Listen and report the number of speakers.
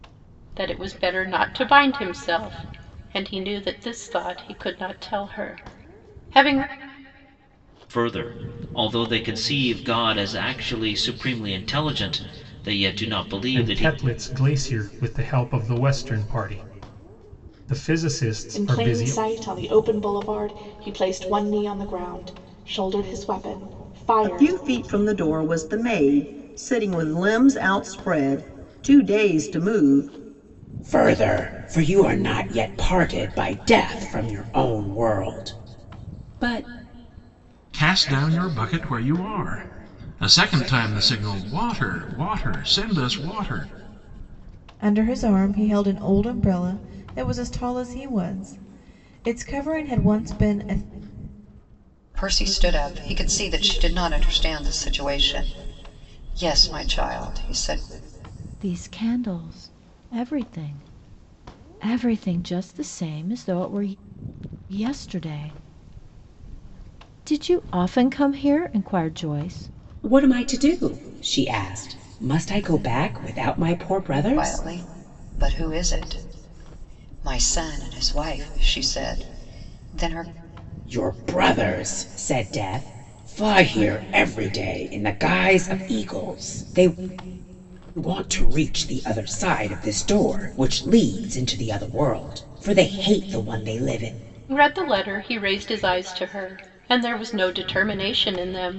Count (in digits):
10